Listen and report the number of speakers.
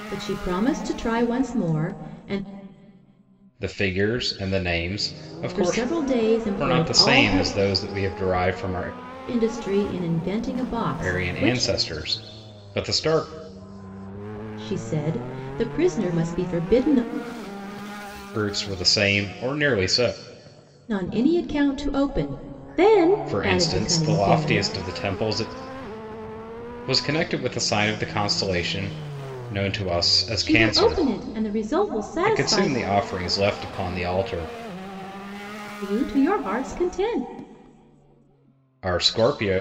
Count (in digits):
2